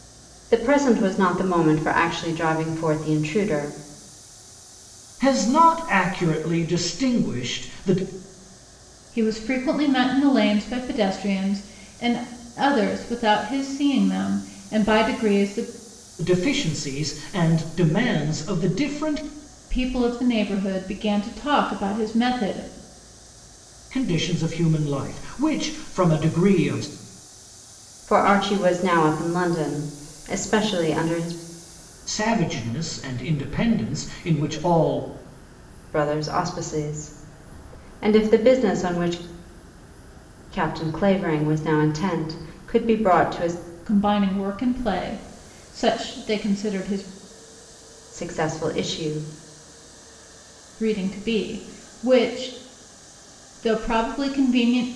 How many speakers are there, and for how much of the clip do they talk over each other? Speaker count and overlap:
3, no overlap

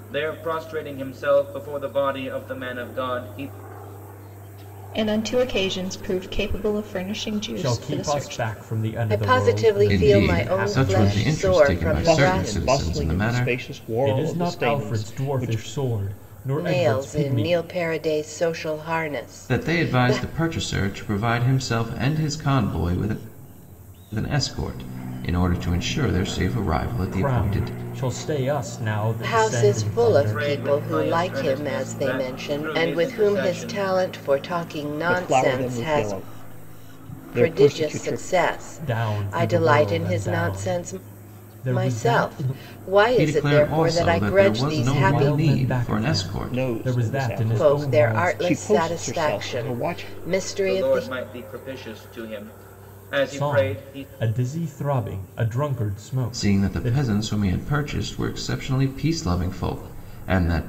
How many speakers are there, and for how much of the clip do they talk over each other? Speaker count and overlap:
6, about 47%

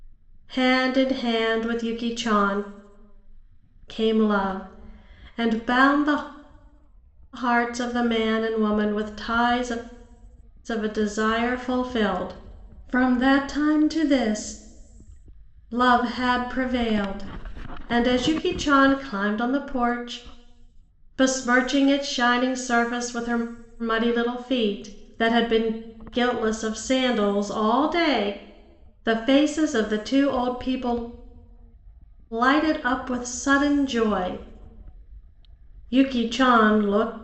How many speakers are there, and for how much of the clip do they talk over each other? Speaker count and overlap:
1, no overlap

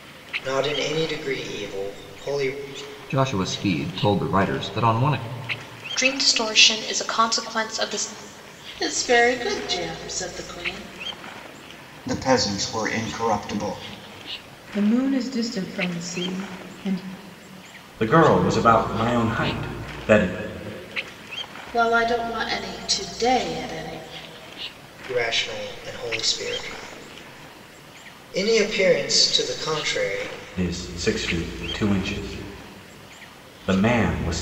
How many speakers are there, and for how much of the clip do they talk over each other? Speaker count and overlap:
7, no overlap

